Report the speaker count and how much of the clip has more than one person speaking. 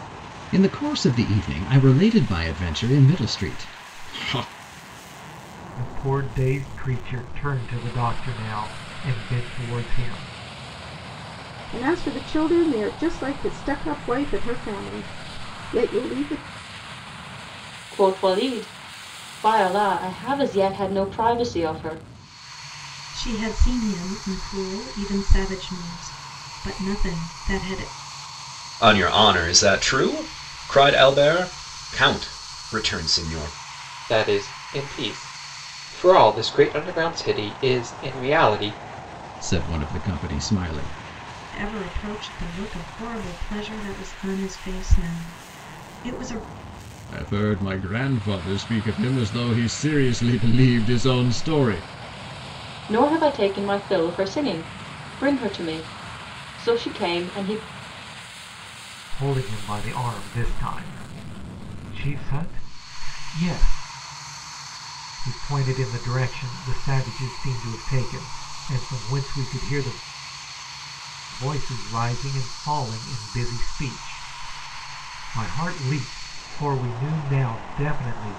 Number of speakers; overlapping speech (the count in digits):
7, no overlap